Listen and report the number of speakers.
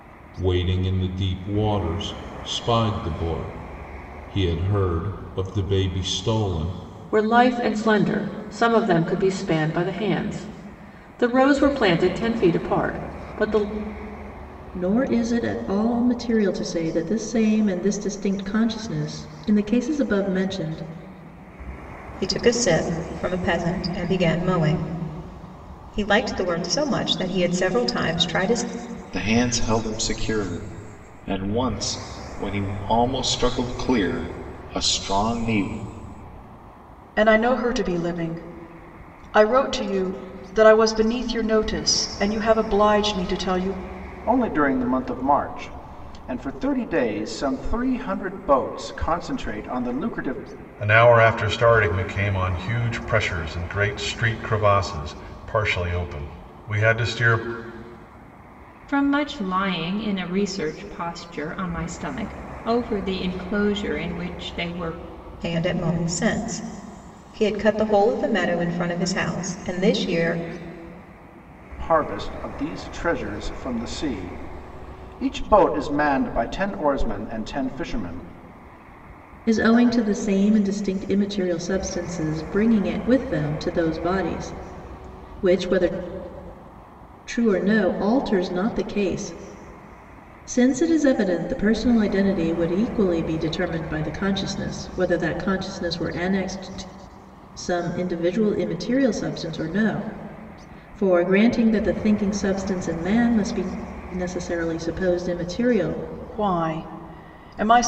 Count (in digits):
9